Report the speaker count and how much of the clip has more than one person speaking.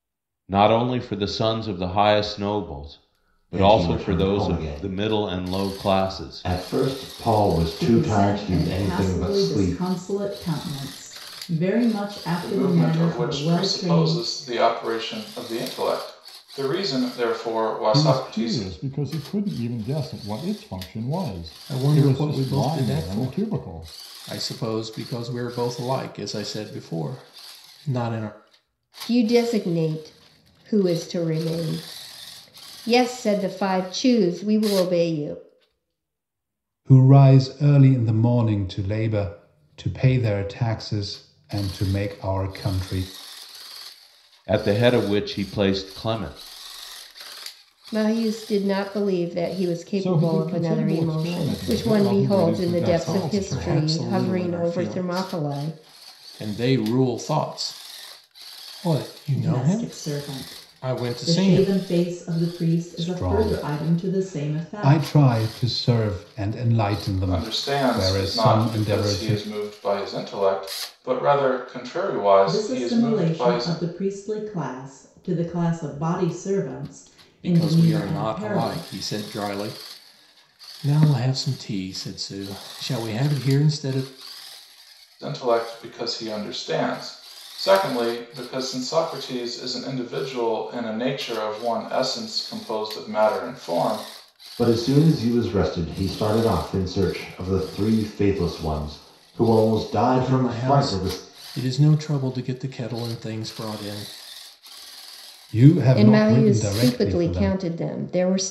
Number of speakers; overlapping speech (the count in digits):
8, about 26%